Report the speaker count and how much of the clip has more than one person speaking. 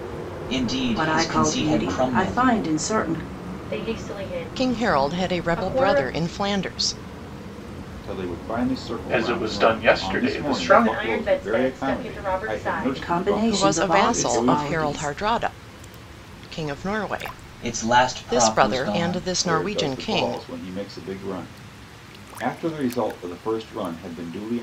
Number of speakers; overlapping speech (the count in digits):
6, about 49%